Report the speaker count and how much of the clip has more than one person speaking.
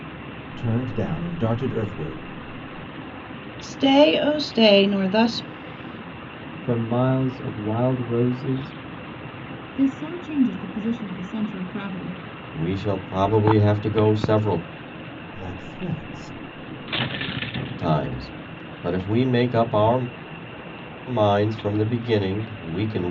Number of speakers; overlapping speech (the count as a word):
five, no overlap